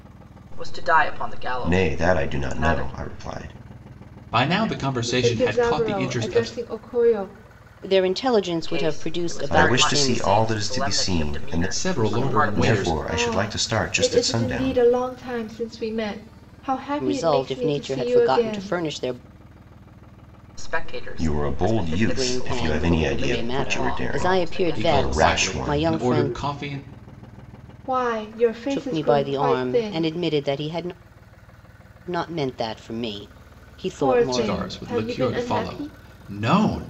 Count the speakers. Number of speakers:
5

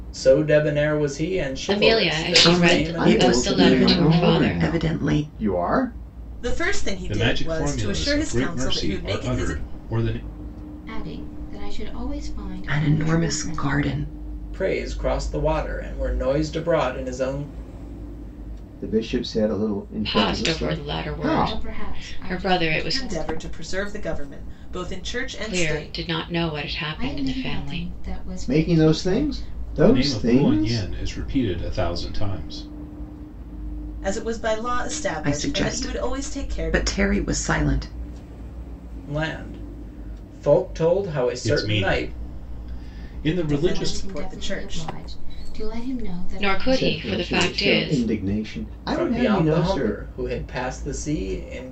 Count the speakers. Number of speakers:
7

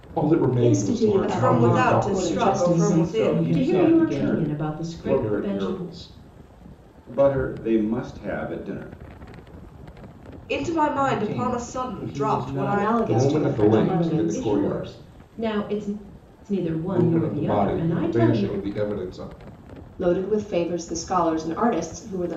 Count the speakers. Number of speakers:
6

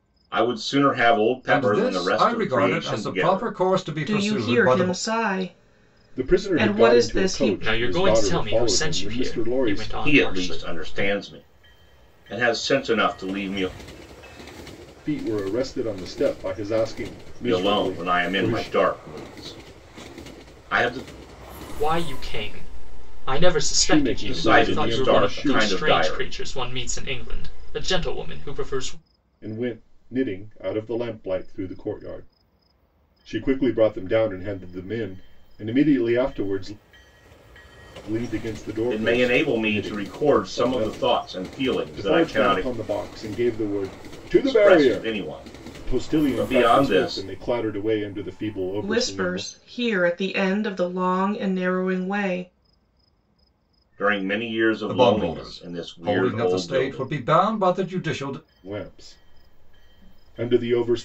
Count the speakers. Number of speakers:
5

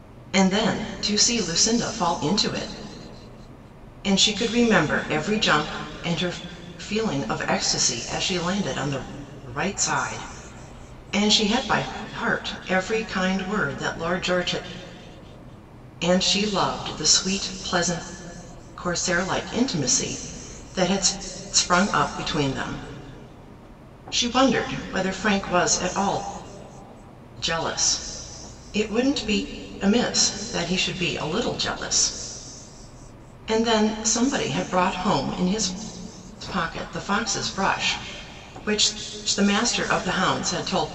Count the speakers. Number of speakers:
1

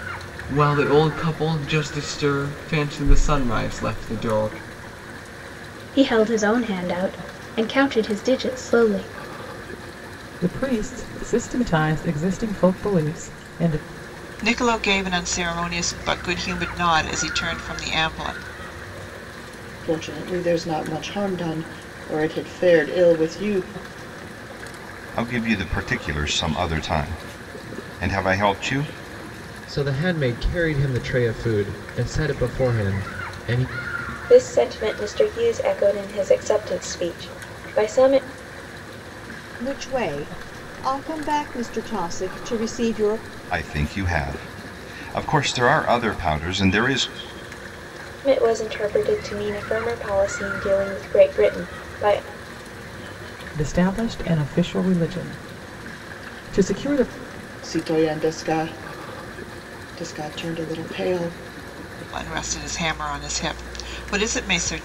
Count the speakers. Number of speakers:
9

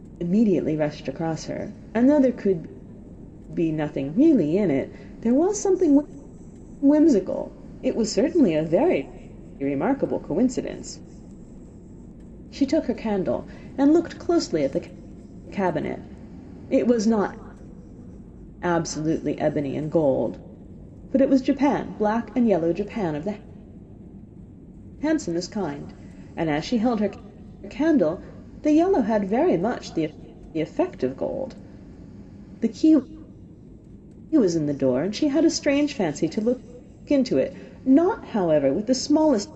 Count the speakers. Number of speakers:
1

